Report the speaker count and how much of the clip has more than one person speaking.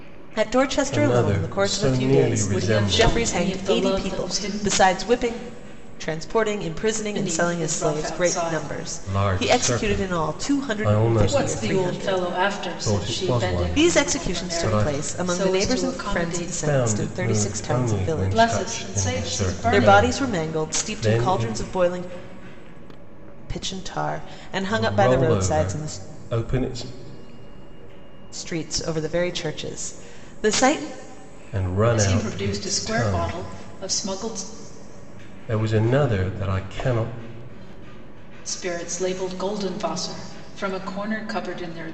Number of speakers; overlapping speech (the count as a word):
three, about 49%